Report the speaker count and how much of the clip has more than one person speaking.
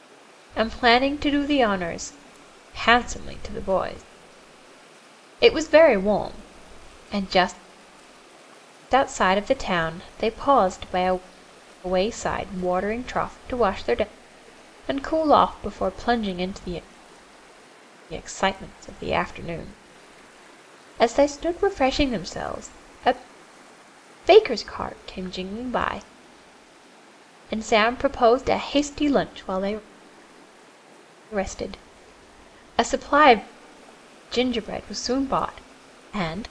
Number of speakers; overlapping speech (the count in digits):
1, no overlap